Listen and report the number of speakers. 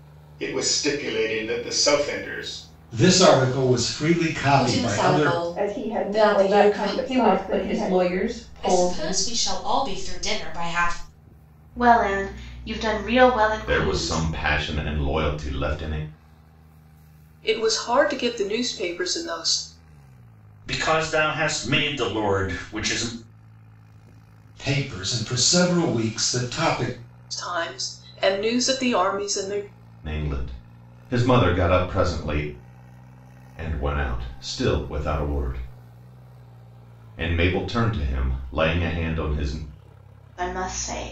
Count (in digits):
10